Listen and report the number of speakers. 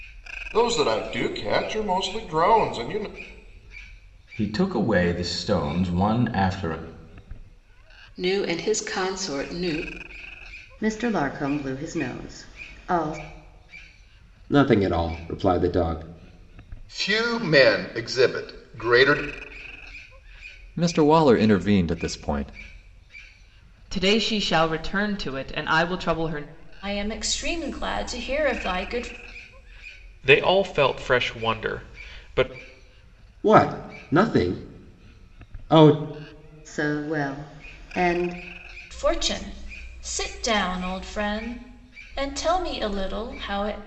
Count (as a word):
ten